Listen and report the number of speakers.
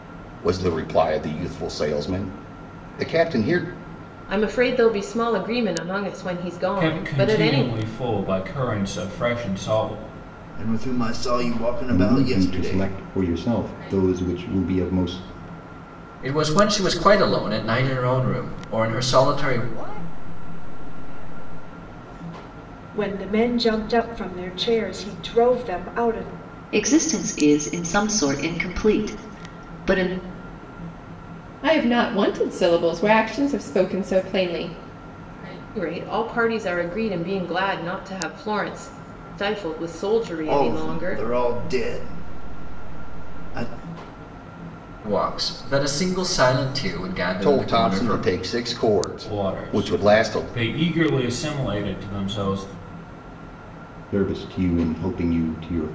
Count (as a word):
ten